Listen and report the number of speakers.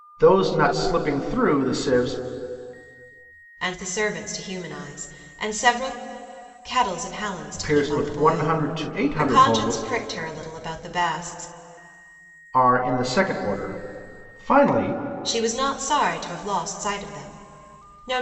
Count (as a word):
two